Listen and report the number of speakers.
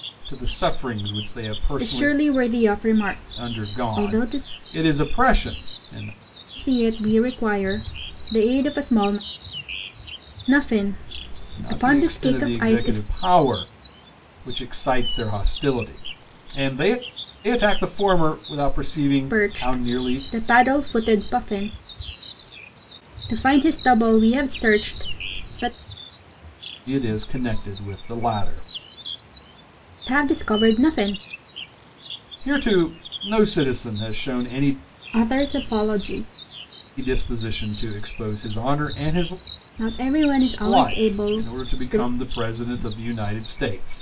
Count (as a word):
two